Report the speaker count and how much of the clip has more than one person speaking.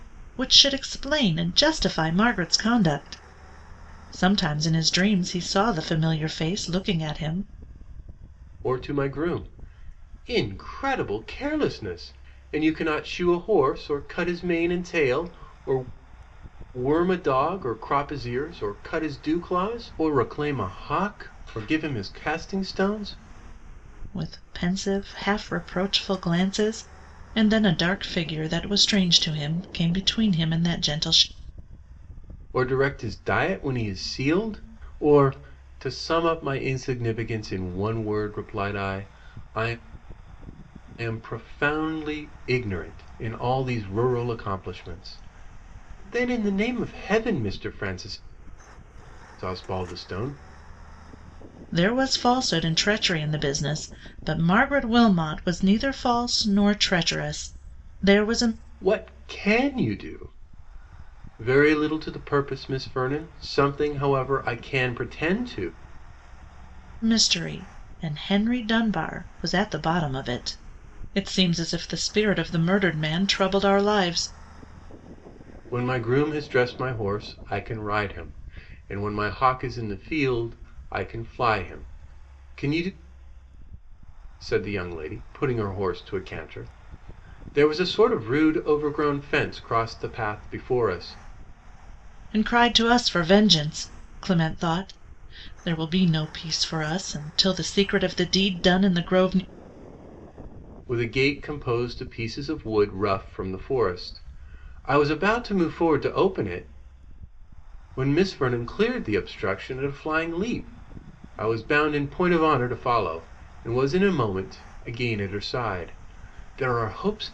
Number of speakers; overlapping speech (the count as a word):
two, no overlap